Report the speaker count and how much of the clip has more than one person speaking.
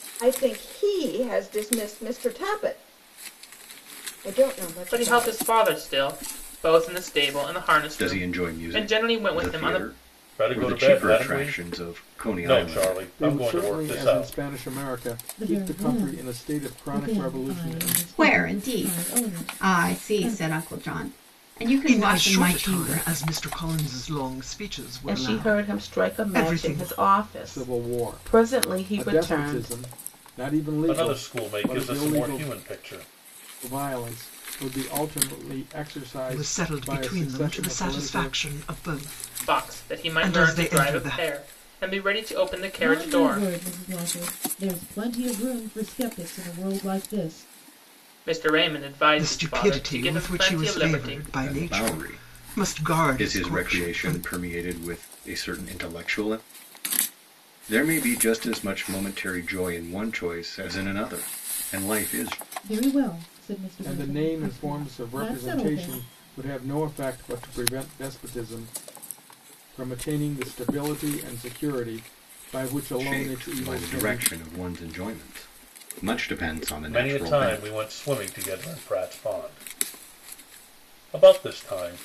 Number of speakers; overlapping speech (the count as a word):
nine, about 40%